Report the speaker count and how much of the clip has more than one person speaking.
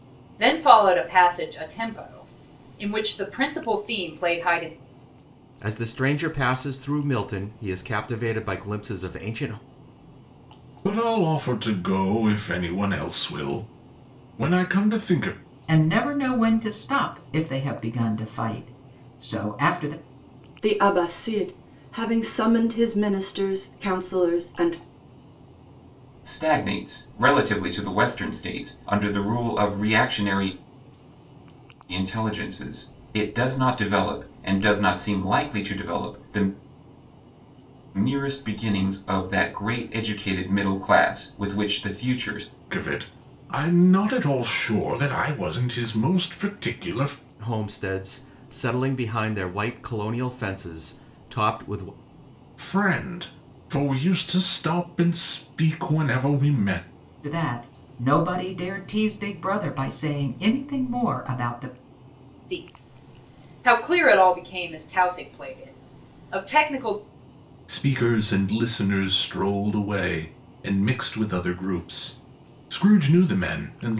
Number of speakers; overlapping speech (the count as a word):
six, no overlap